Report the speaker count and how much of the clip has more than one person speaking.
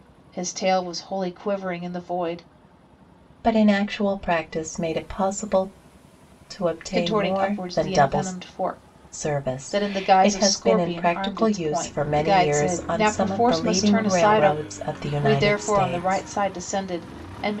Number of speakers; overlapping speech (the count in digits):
2, about 43%